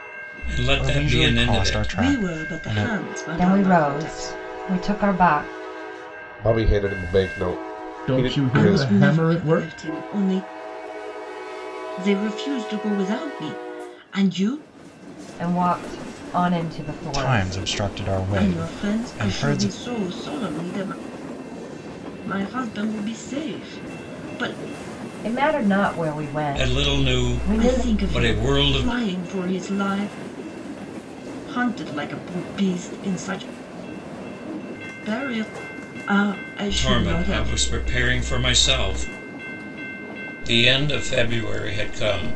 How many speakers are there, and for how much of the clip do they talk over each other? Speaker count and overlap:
six, about 25%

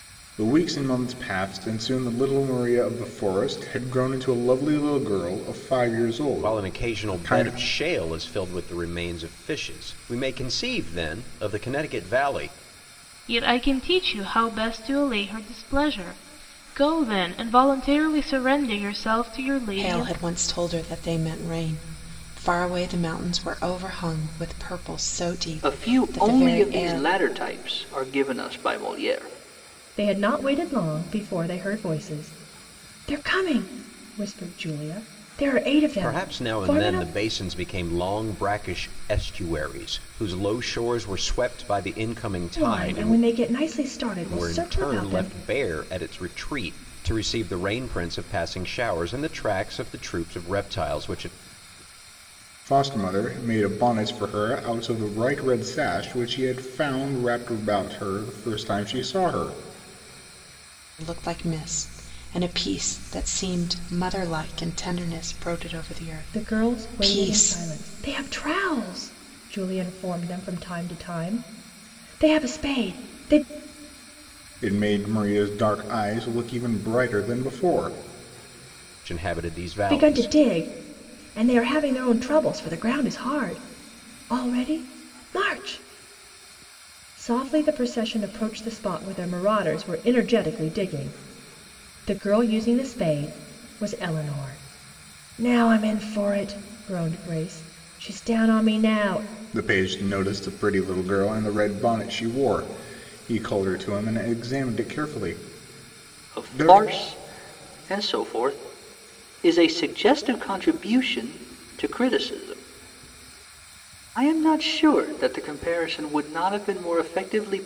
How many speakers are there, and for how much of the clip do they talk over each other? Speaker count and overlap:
six, about 7%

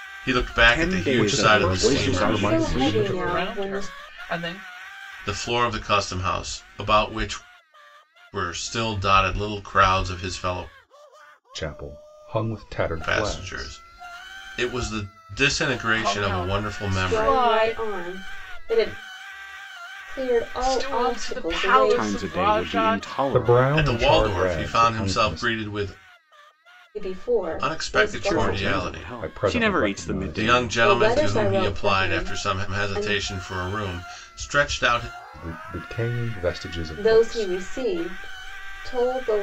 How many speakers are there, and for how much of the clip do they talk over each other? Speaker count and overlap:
five, about 42%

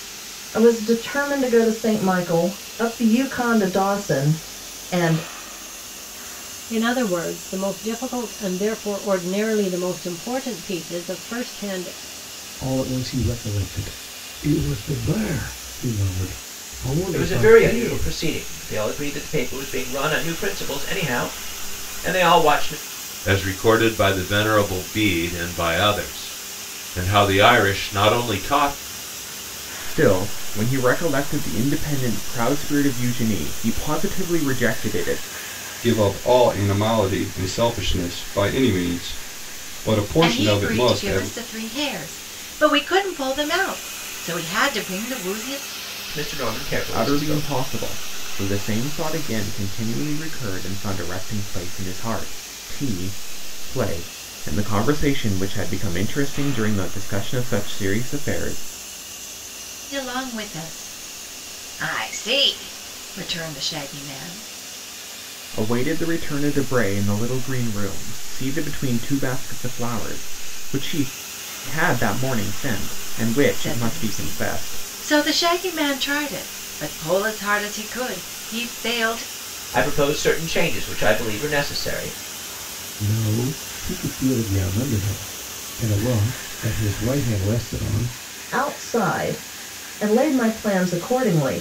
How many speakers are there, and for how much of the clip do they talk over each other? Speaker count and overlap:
eight, about 5%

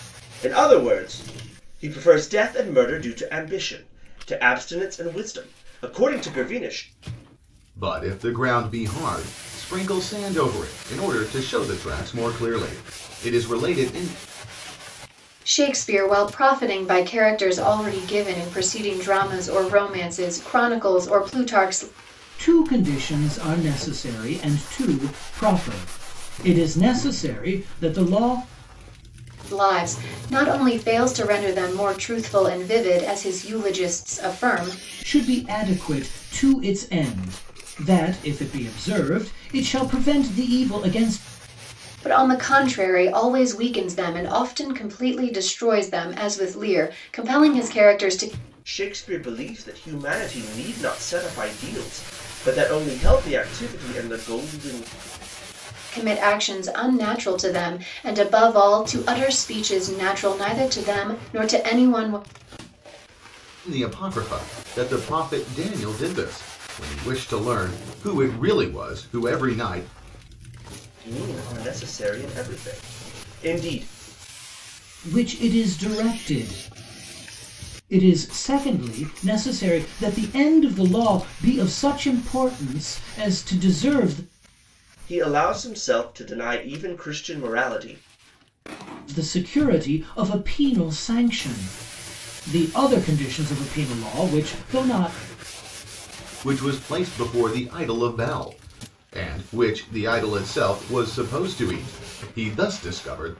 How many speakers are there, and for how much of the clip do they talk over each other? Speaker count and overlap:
four, no overlap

